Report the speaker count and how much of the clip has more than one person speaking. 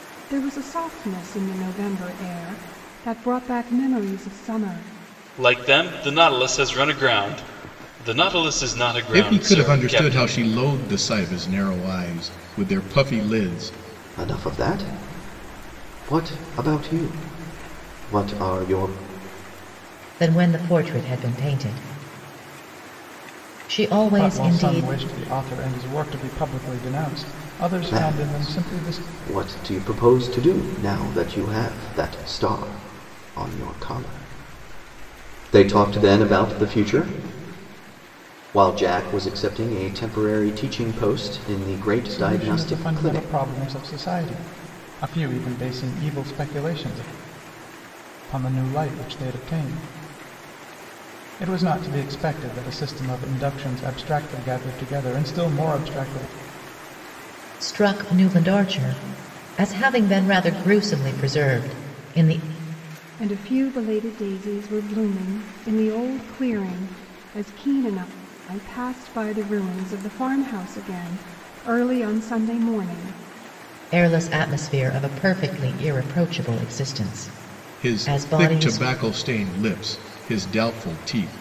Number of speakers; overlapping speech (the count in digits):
6, about 7%